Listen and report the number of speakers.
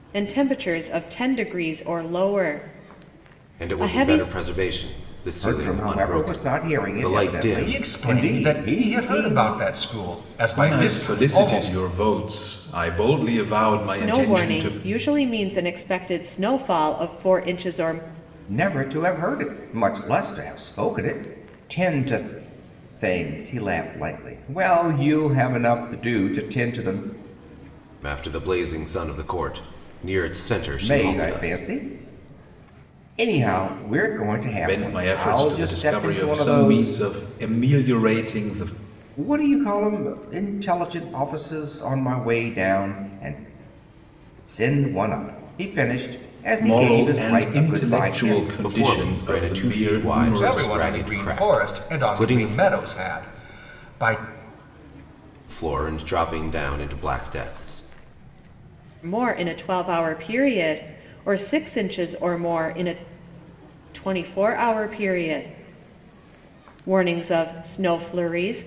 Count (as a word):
five